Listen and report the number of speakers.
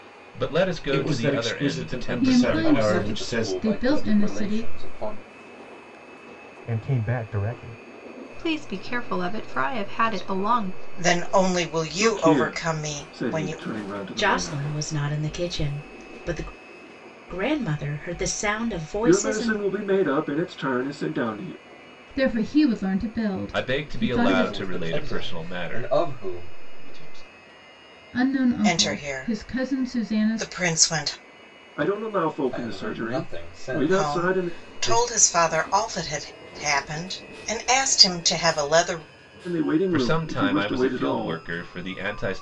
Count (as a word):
ten